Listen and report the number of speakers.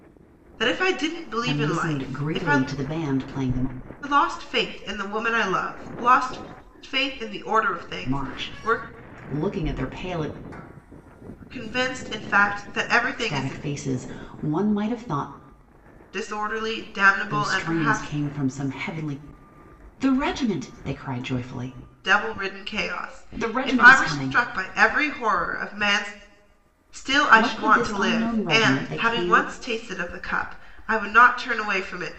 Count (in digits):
2